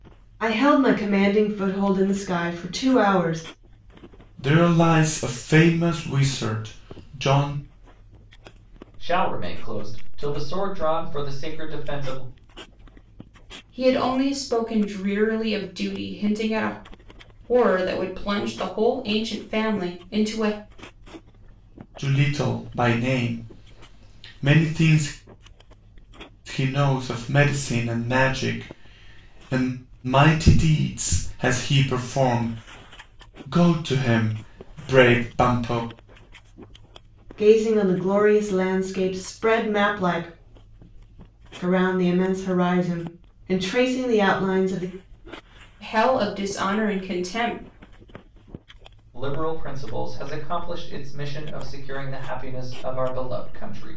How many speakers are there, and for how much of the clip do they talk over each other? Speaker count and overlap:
4, no overlap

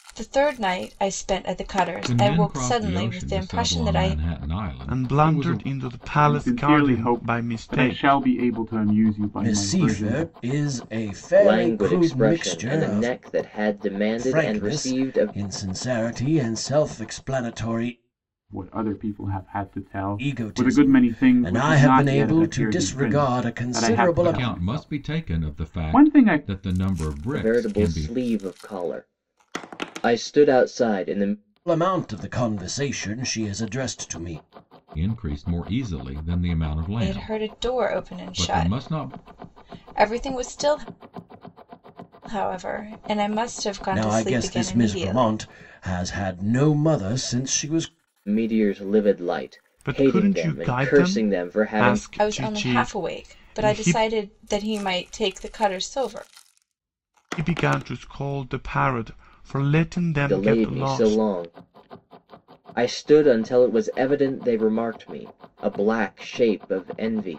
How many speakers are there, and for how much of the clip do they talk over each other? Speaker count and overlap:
6, about 37%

